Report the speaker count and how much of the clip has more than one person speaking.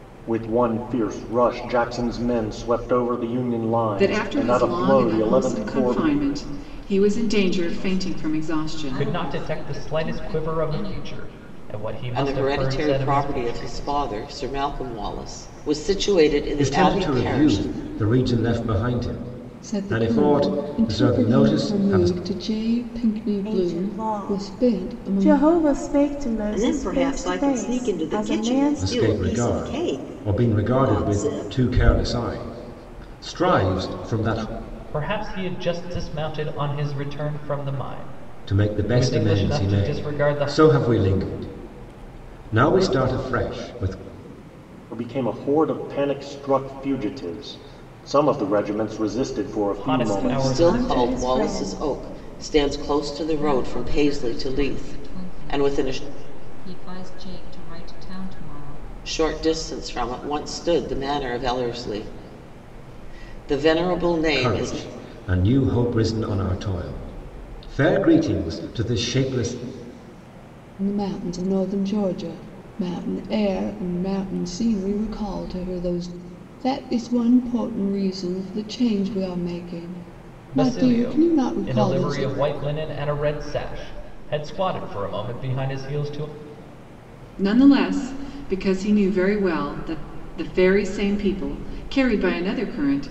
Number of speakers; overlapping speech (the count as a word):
nine, about 31%